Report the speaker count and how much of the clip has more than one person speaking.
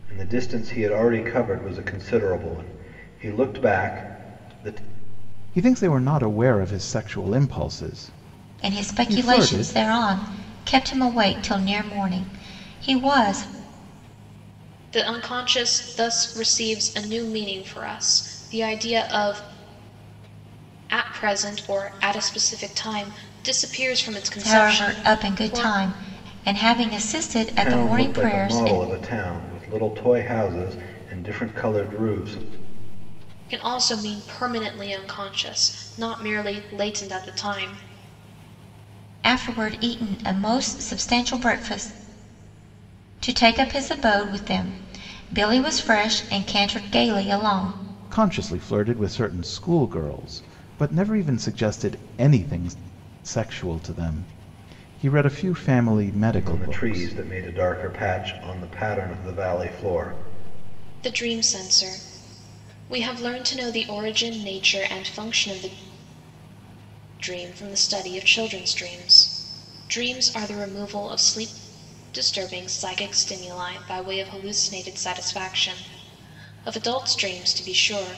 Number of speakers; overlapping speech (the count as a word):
four, about 6%